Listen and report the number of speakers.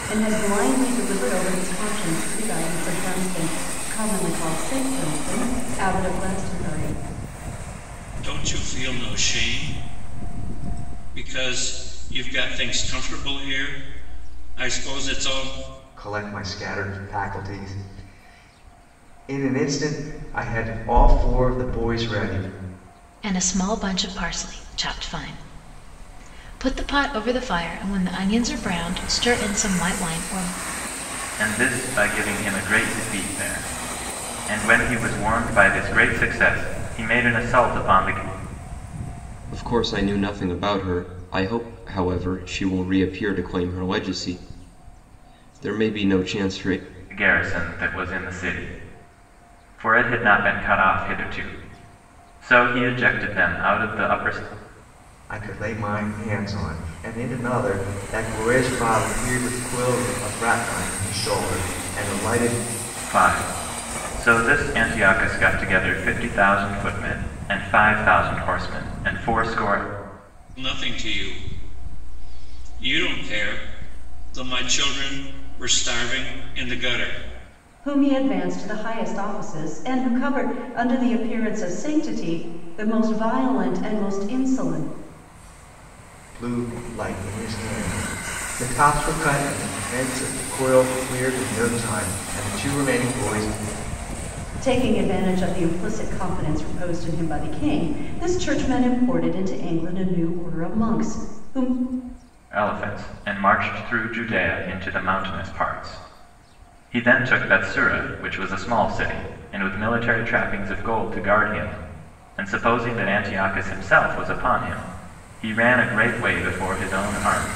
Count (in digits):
6